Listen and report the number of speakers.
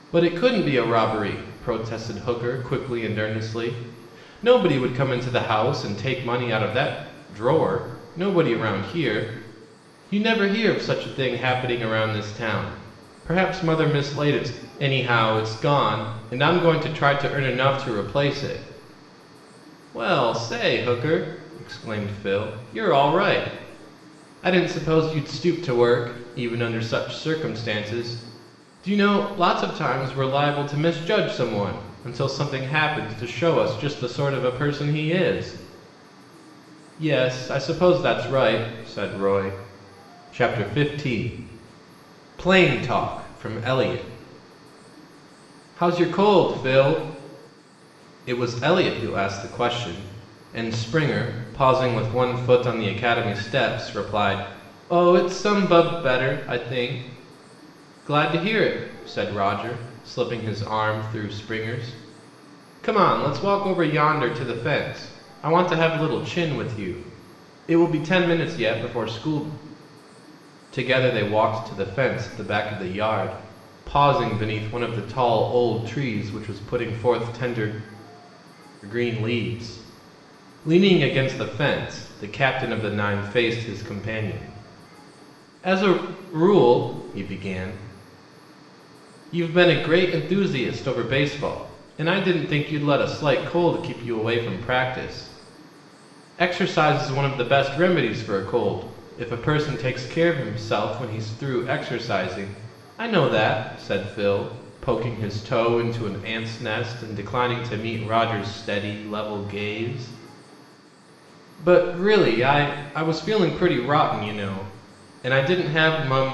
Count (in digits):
1